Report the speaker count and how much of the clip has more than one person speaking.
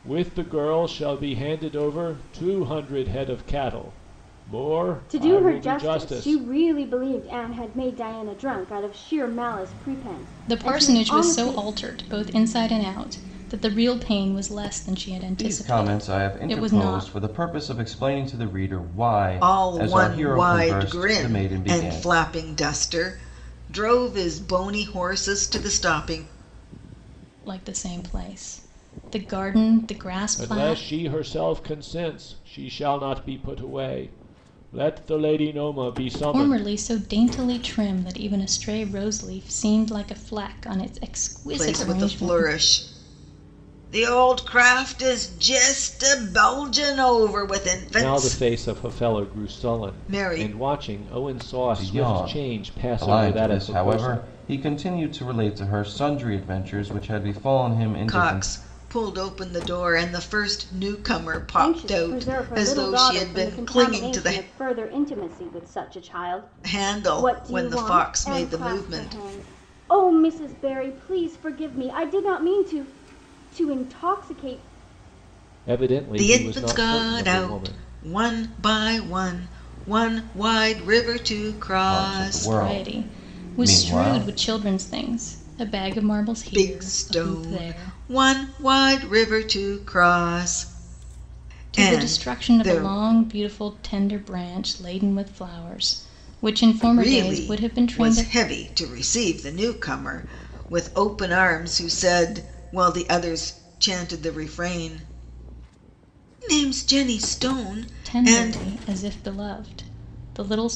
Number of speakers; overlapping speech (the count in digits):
5, about 27%